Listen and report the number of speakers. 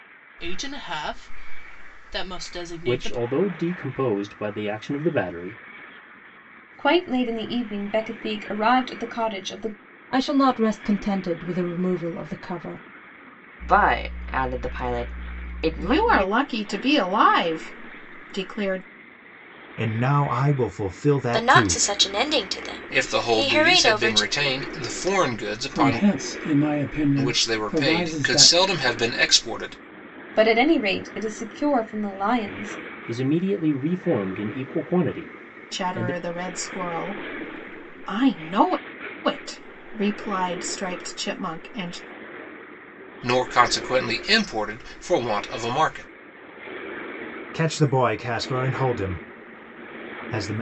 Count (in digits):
10